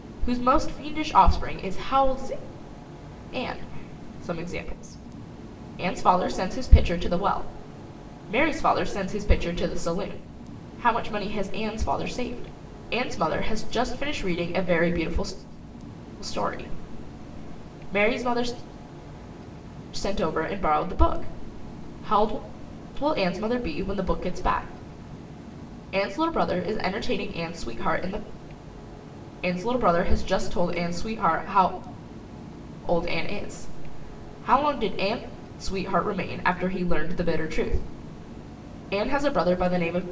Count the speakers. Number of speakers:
one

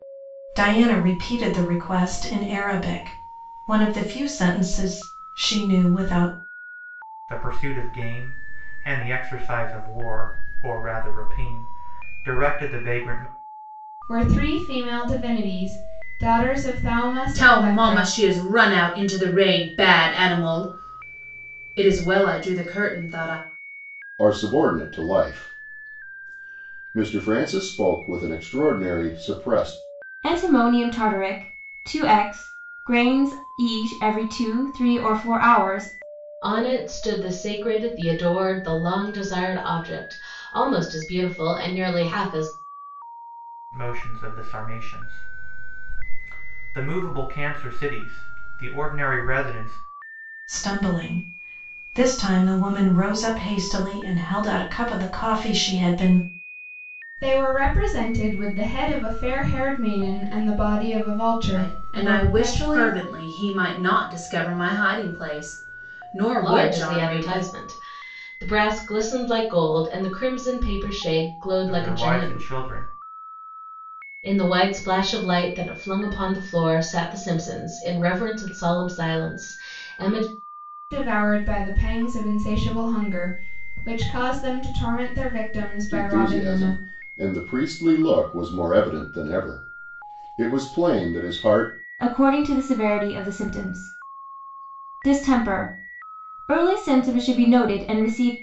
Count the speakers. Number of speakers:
seven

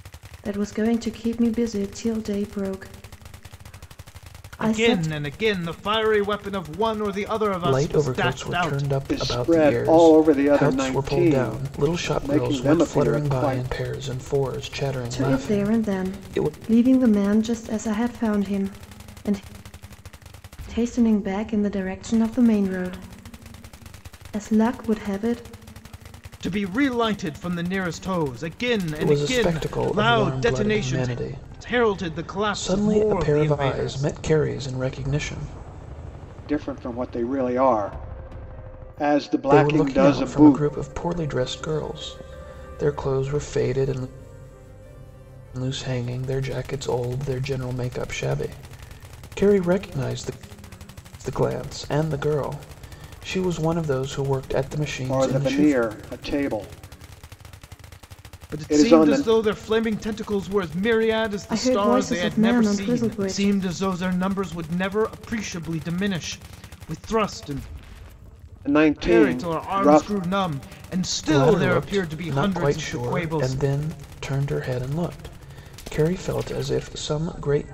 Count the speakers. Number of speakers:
four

